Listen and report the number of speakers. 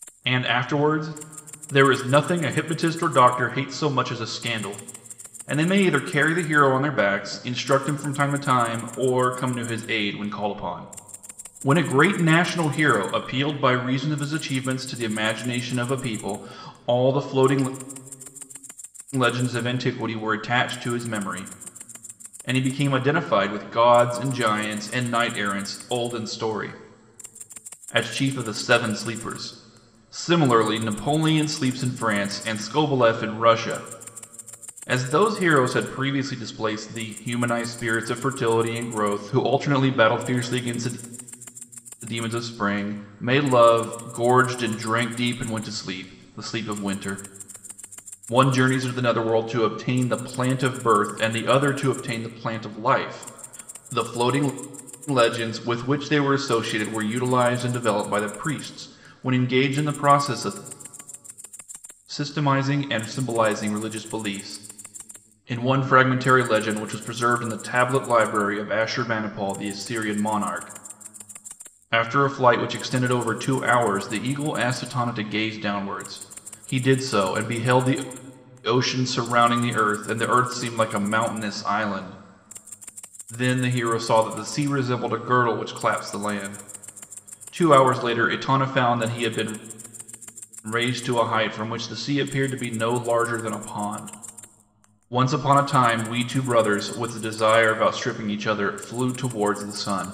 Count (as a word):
one